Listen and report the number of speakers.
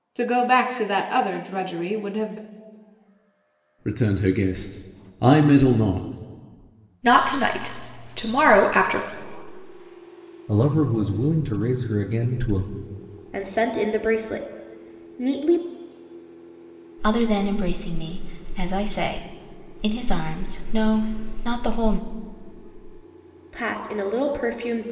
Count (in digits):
6